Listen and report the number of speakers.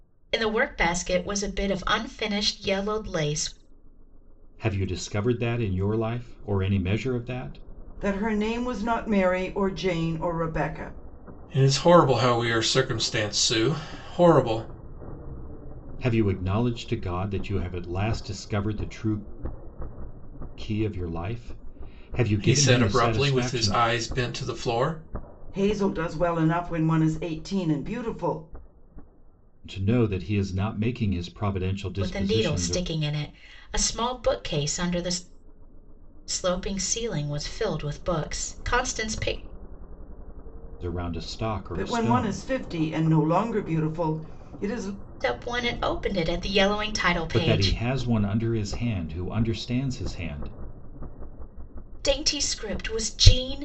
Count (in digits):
4